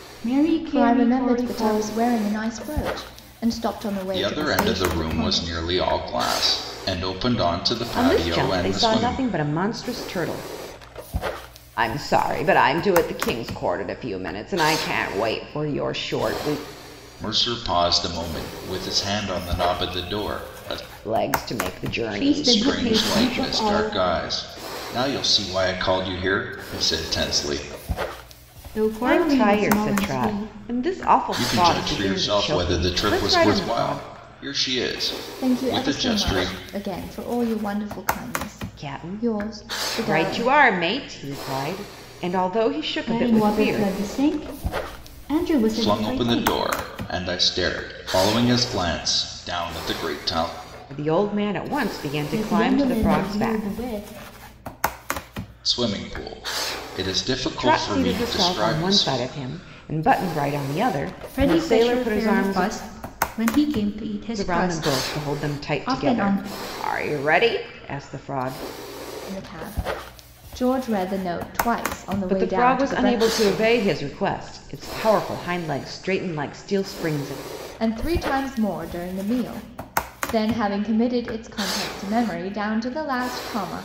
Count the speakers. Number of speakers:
4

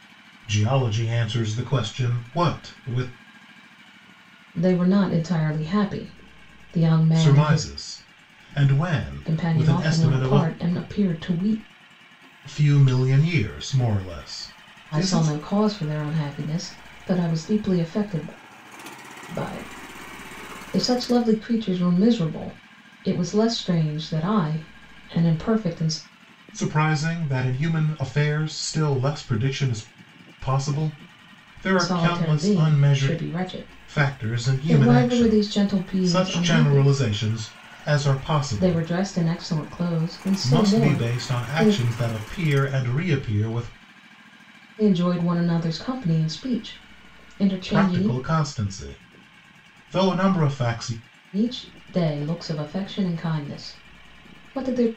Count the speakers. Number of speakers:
2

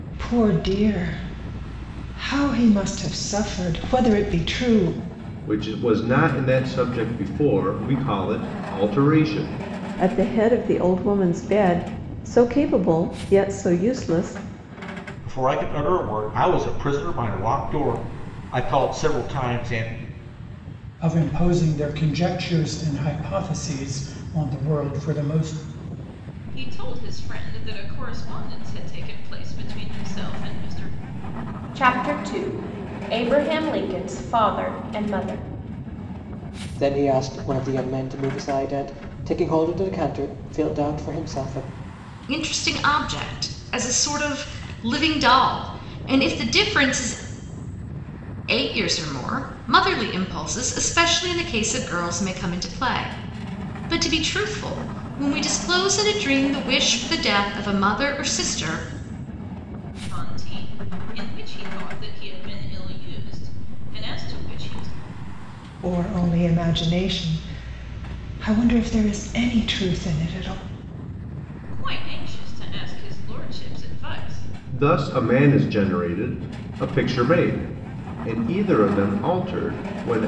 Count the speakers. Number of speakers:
9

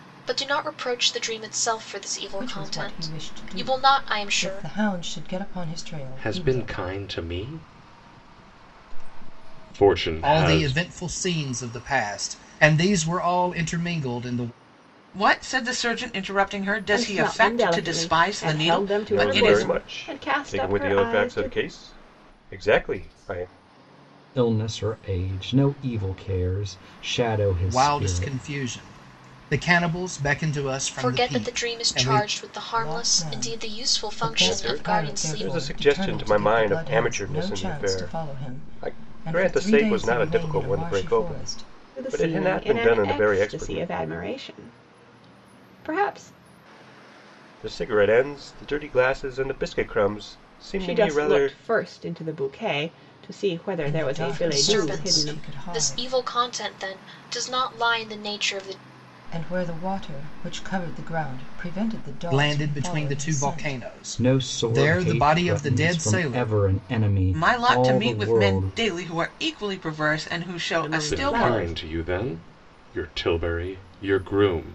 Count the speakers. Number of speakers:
8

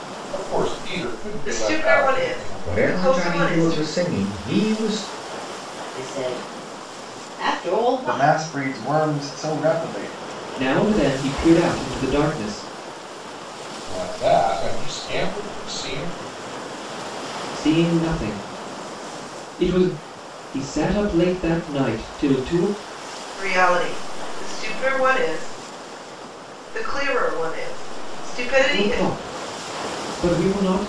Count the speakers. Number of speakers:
6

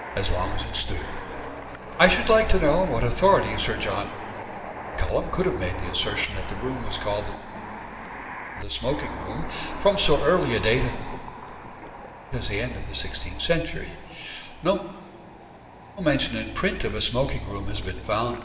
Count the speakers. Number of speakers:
1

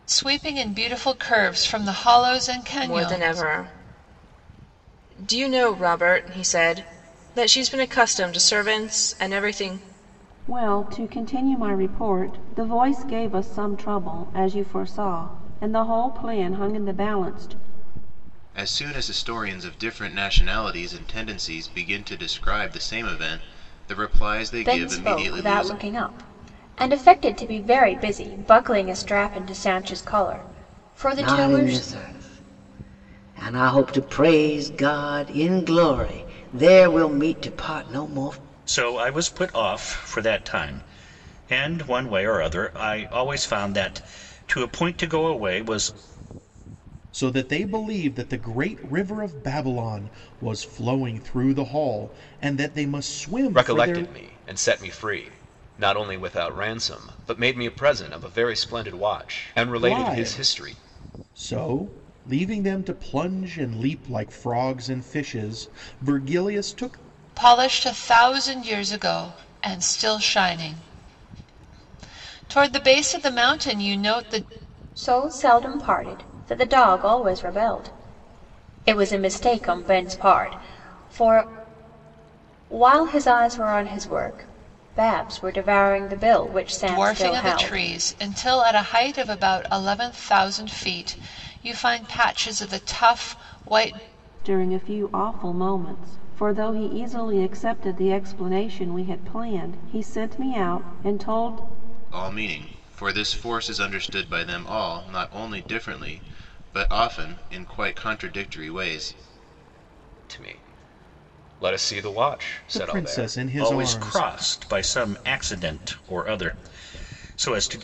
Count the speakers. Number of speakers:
9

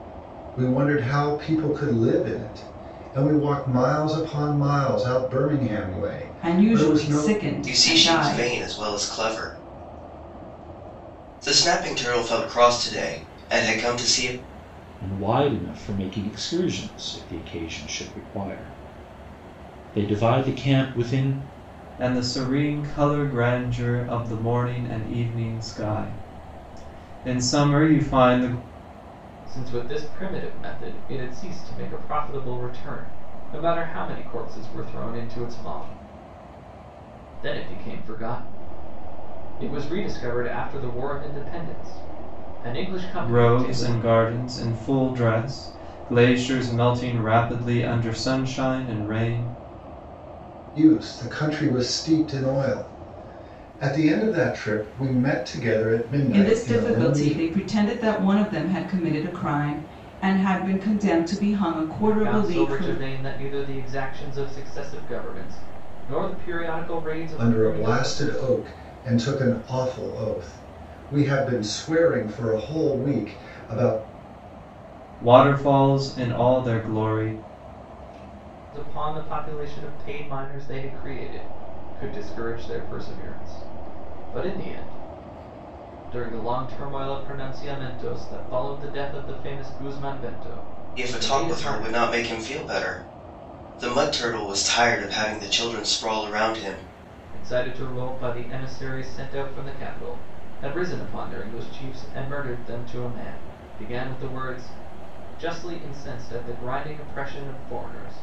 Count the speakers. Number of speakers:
6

